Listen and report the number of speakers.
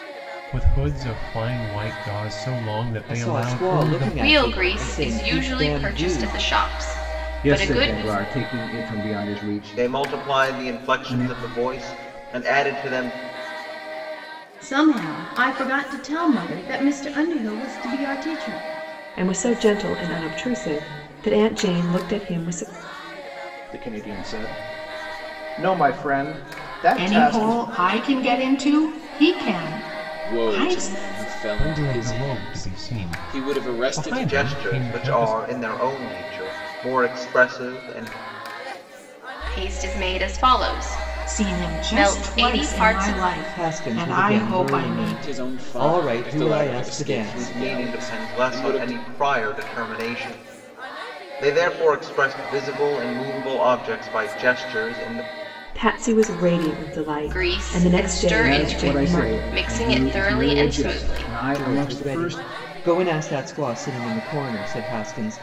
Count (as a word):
ten